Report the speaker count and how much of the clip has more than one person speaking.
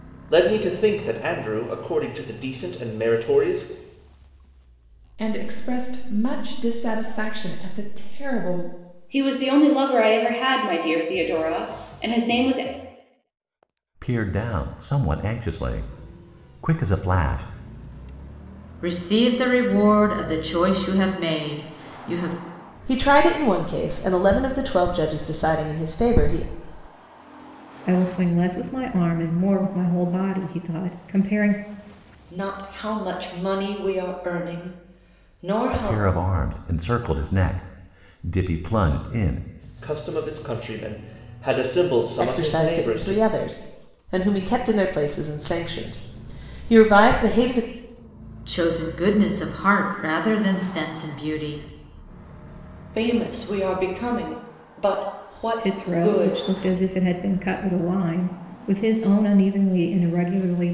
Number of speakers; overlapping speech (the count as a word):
eight, about 4%